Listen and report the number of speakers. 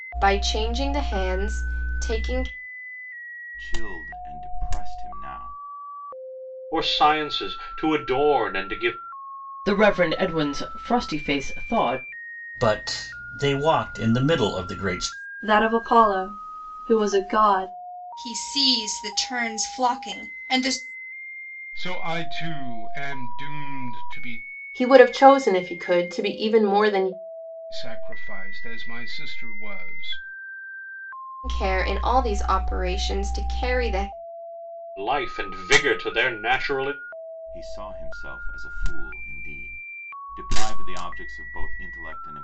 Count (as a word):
nine